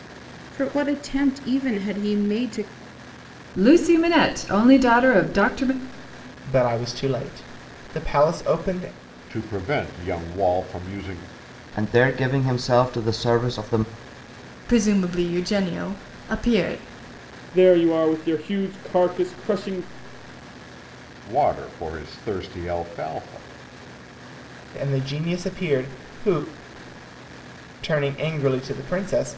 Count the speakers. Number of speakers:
7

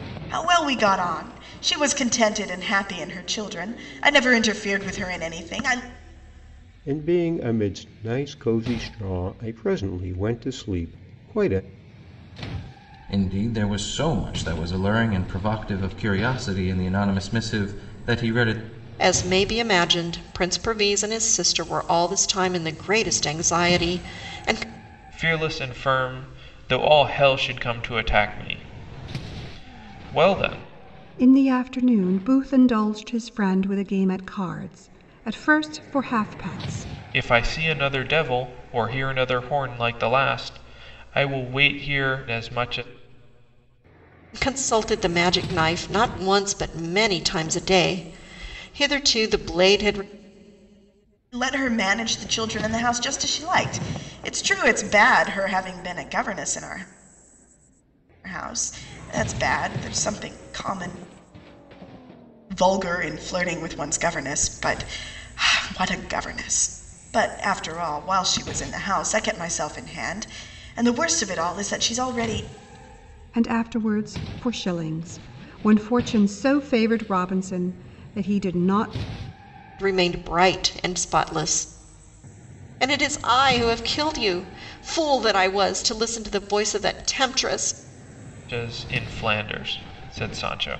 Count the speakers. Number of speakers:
6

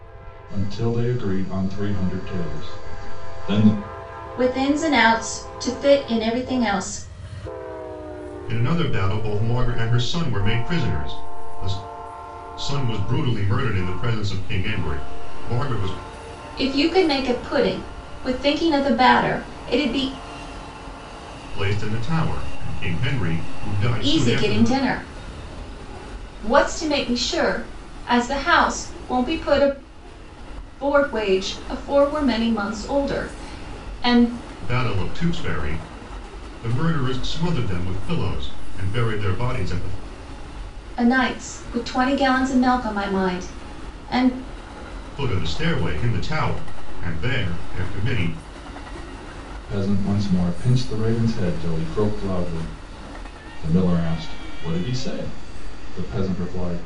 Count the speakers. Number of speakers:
3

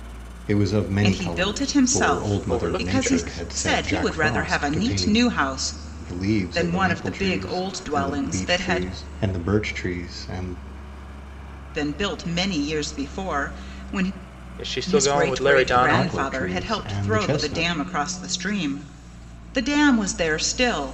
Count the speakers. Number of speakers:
3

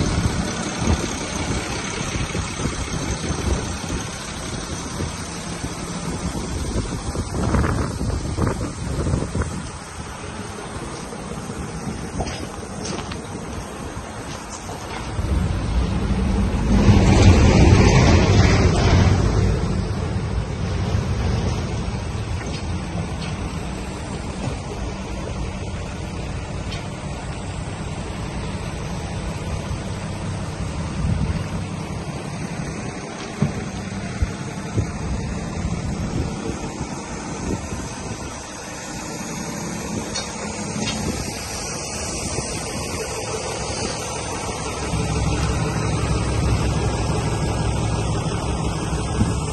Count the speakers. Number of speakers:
0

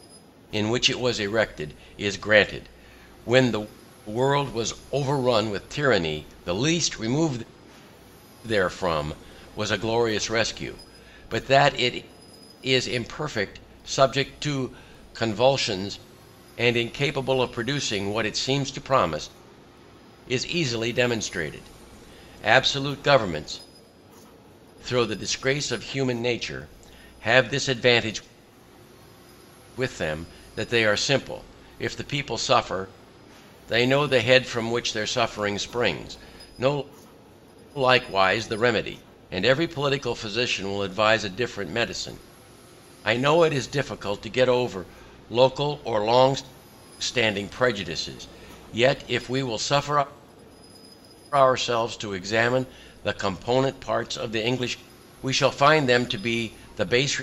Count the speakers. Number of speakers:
1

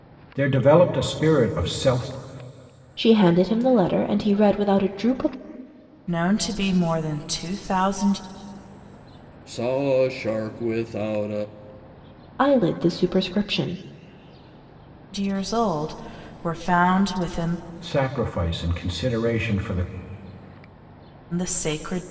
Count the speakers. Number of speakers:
4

